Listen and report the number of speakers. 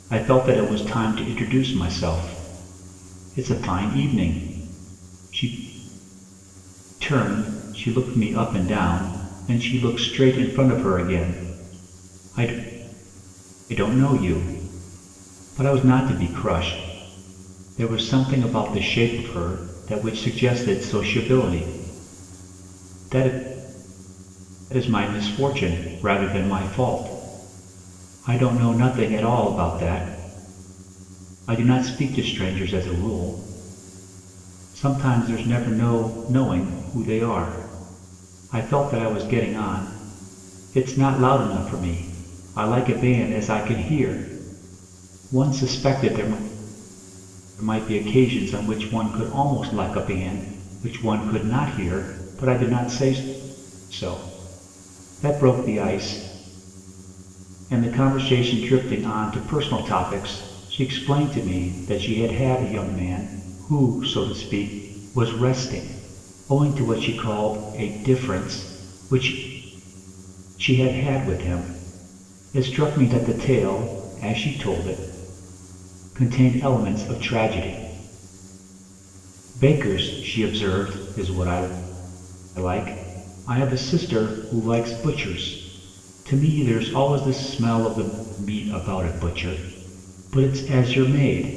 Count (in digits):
1